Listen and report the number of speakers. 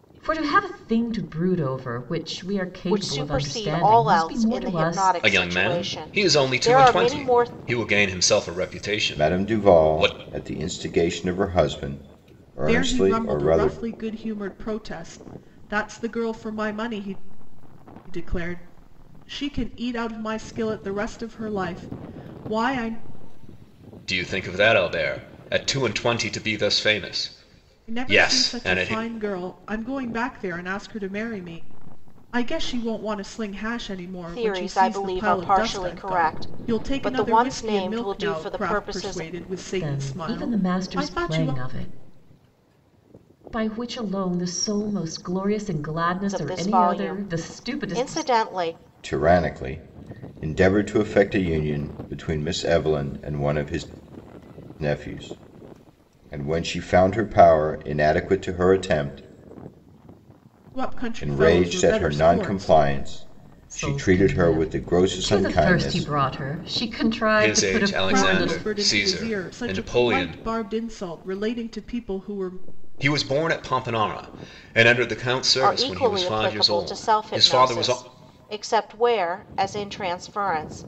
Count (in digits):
5